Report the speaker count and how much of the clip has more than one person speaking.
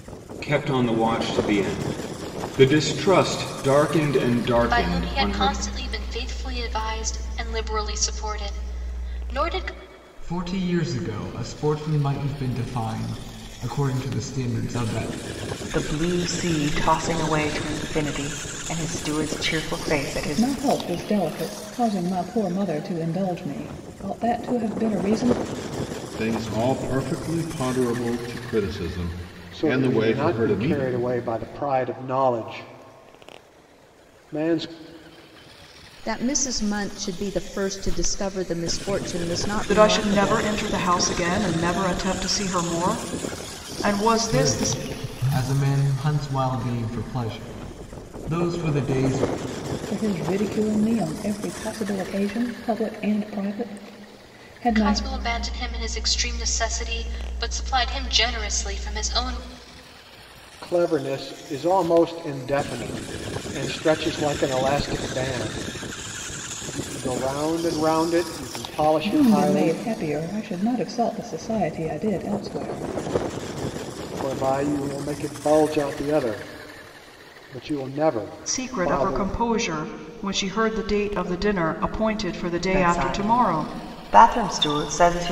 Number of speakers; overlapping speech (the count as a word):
nine, about 8%